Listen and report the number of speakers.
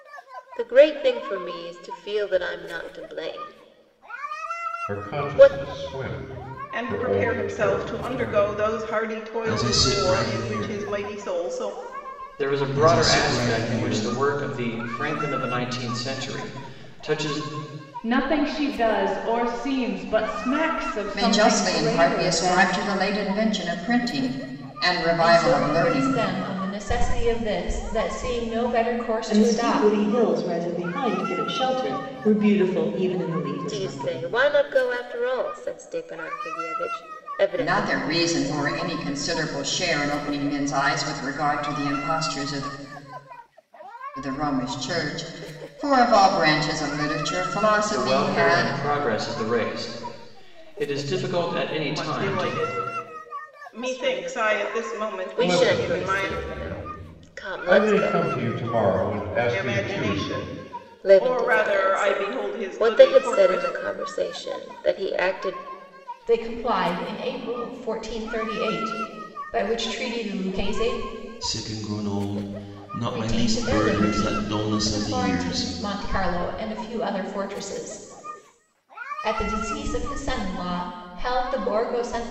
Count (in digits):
9